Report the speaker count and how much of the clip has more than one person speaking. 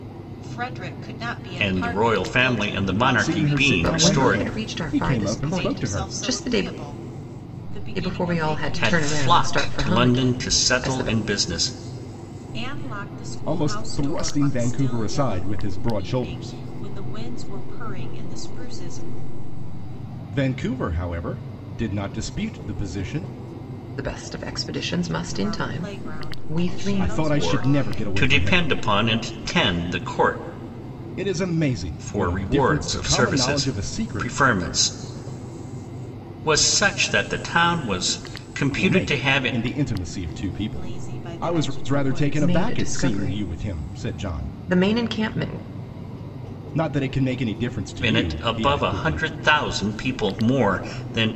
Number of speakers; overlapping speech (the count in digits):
4, about 44%